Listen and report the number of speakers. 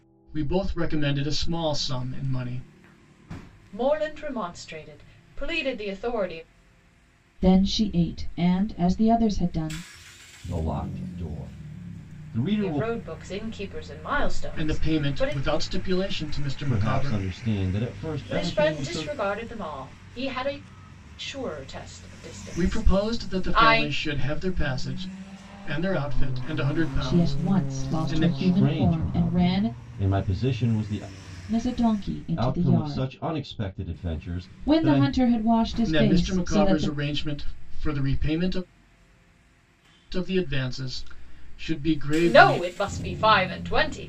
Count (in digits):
4